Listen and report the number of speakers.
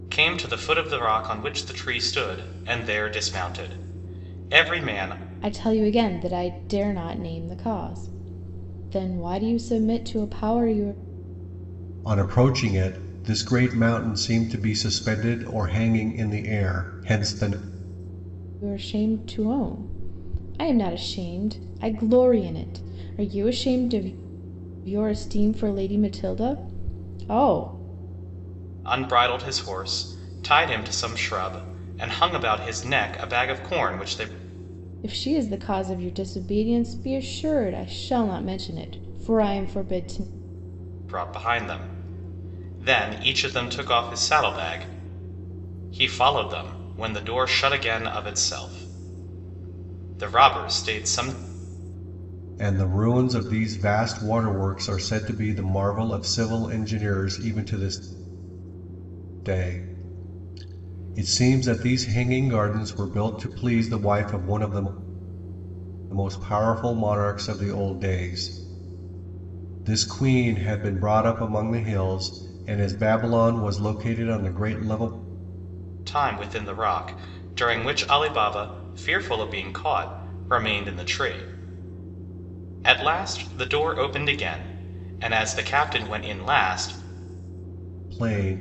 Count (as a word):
three